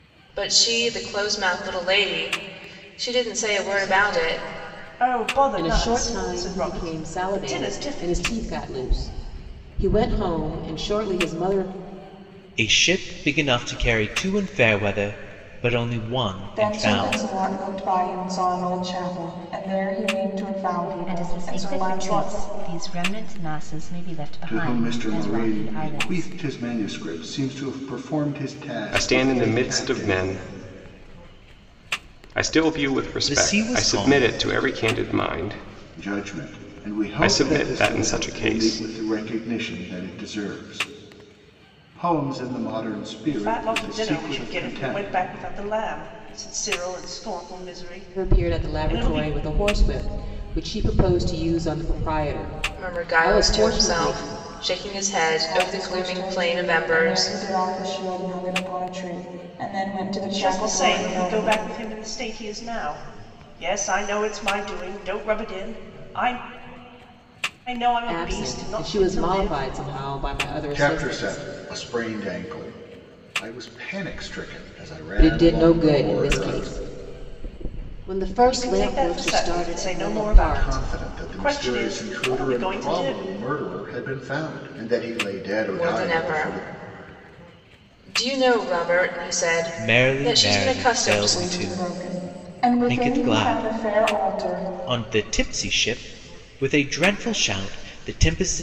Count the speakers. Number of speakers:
8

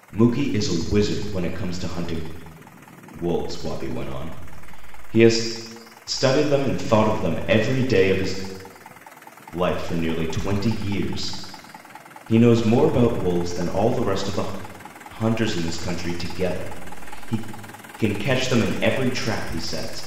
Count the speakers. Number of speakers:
1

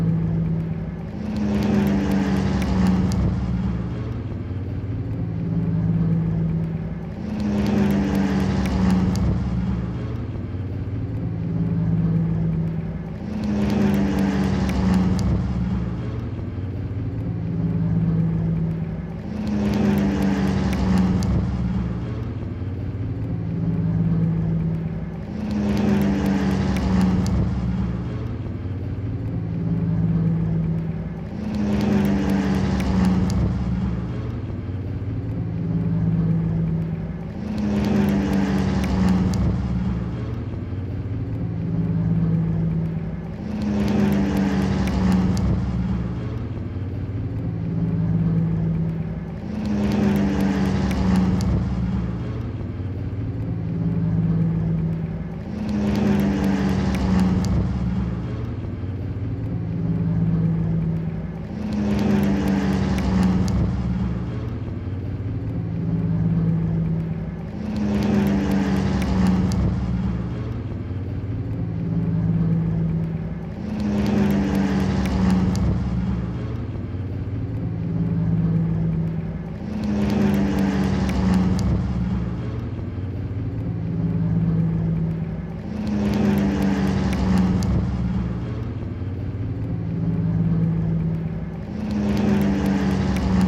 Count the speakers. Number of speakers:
0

